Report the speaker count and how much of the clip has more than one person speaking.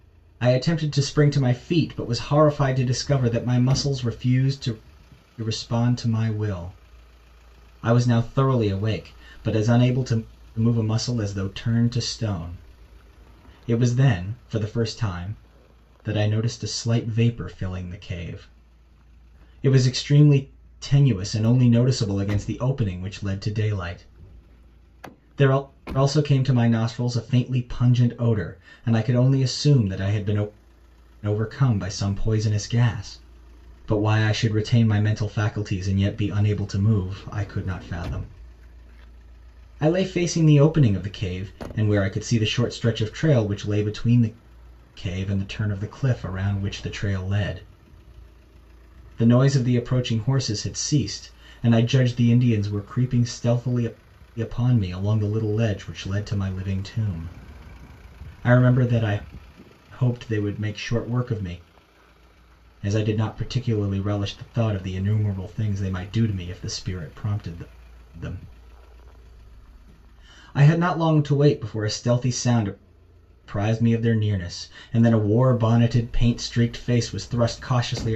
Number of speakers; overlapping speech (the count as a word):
one, no overlap